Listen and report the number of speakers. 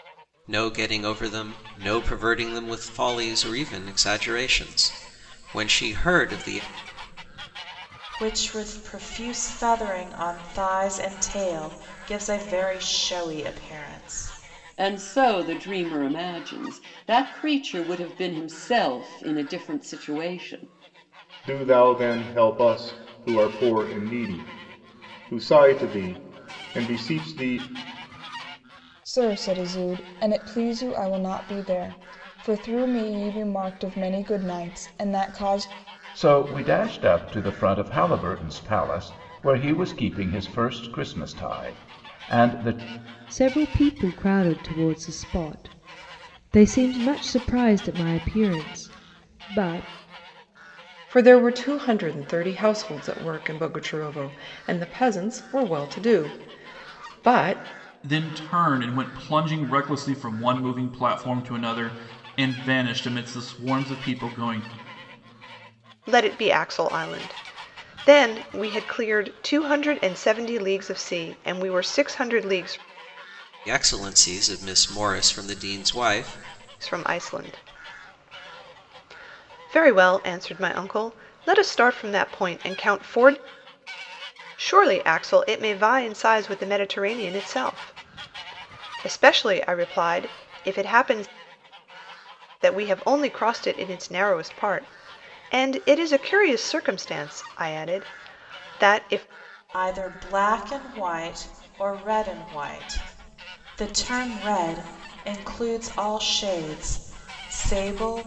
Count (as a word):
ten